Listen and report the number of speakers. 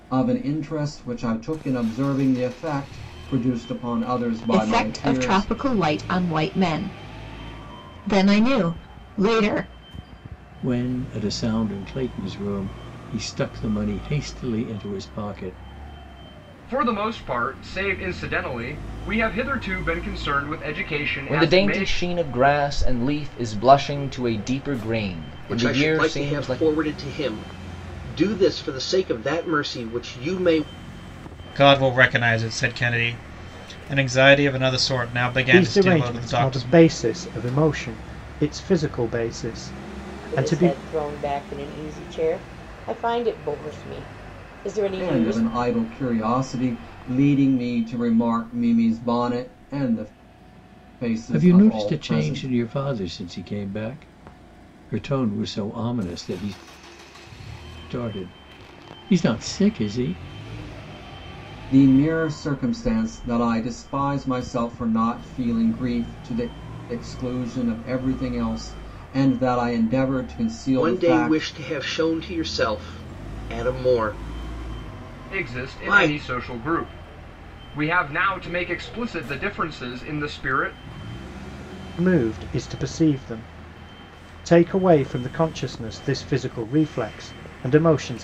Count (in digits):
9